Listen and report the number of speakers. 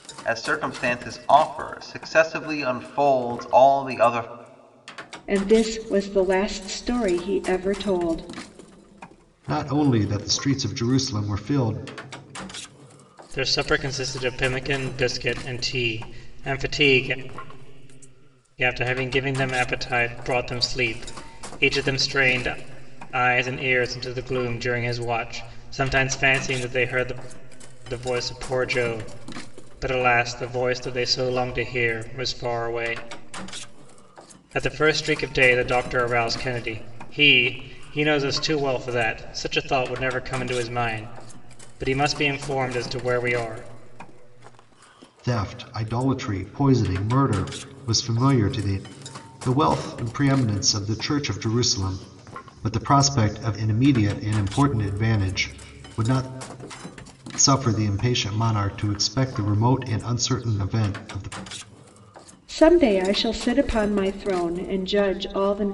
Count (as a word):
four